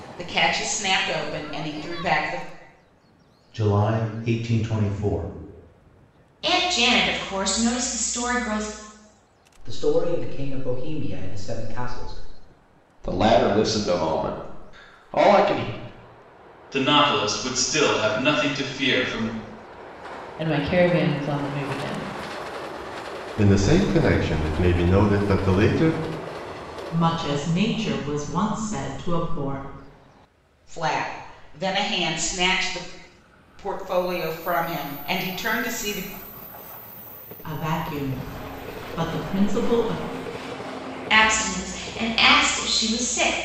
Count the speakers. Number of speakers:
9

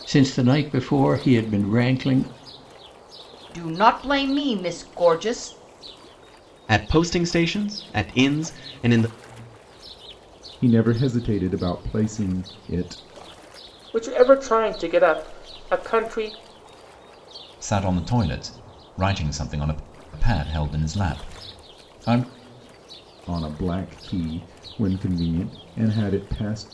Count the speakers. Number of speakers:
6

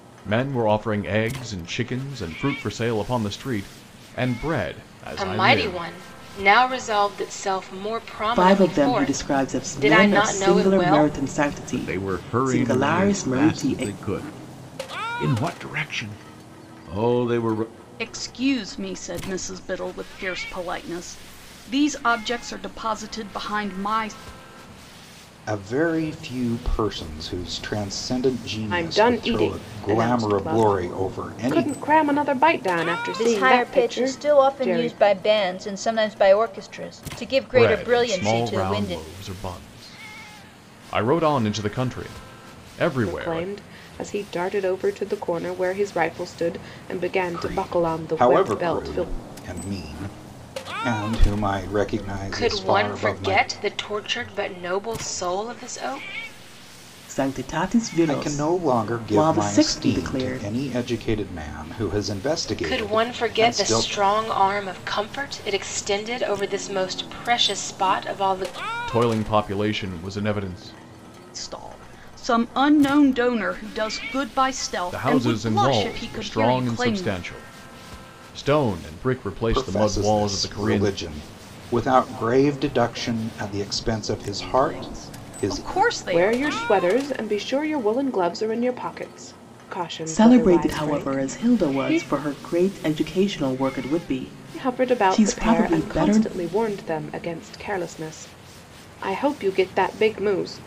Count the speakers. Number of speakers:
8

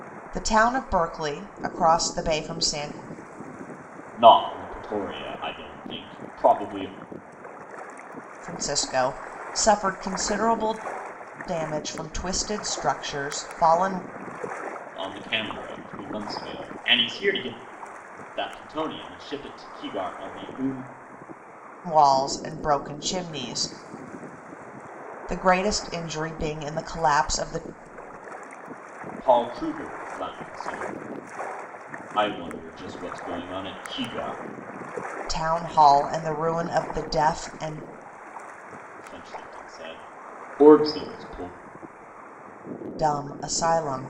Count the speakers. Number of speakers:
2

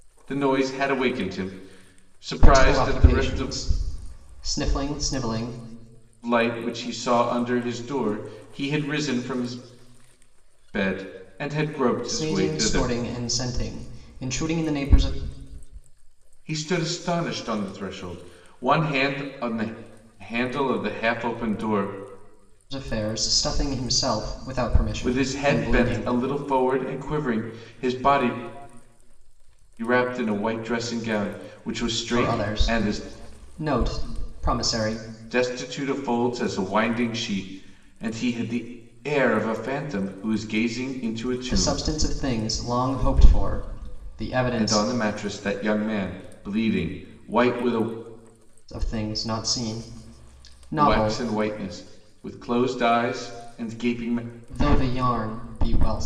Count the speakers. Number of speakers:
2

